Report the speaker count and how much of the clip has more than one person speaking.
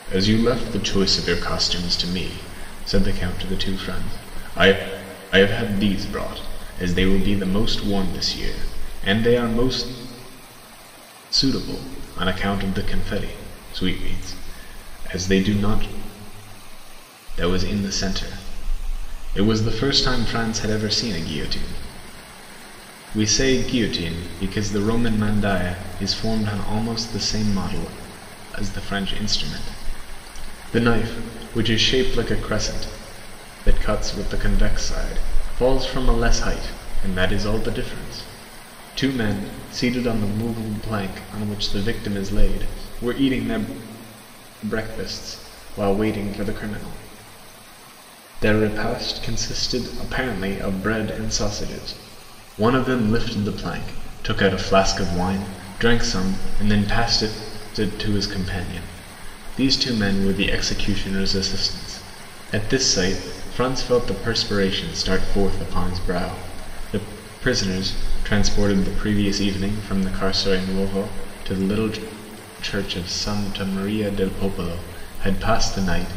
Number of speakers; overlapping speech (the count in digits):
1, no overlap